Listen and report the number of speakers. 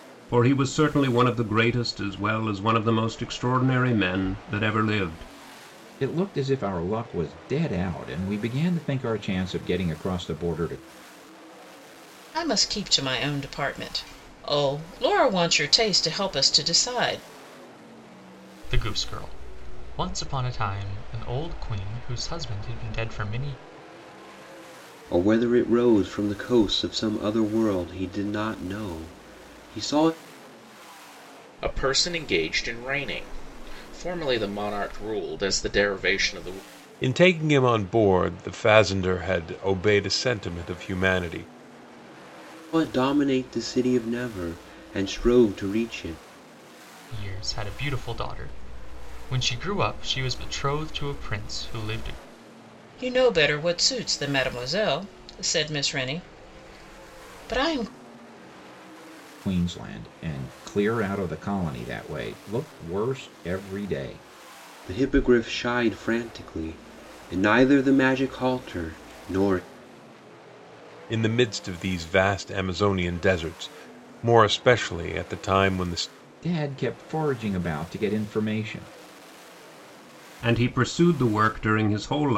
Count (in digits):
7